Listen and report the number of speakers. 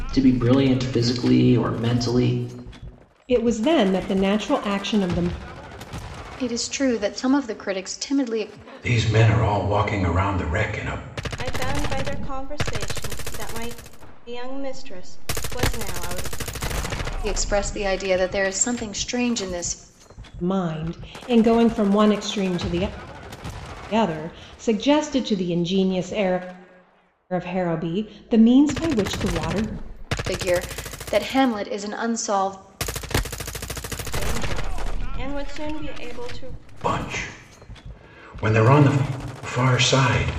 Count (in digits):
5